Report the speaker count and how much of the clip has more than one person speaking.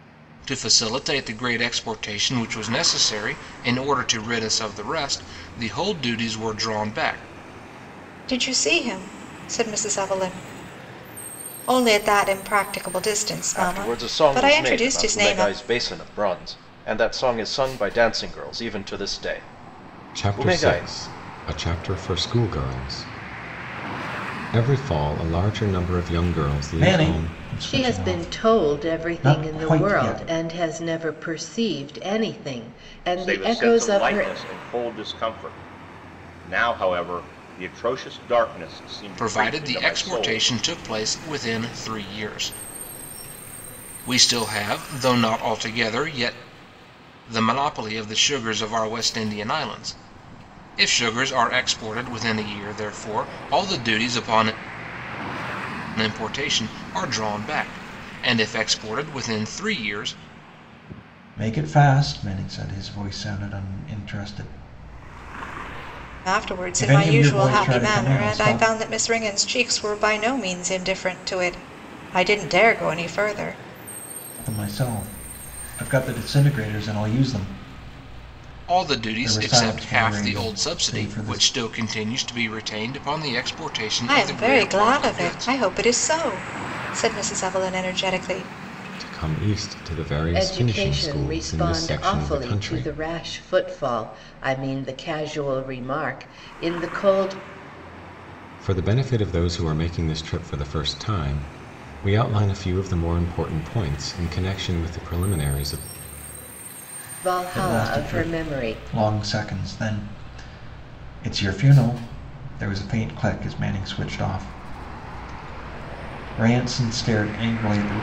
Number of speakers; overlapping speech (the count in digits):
7, about 16%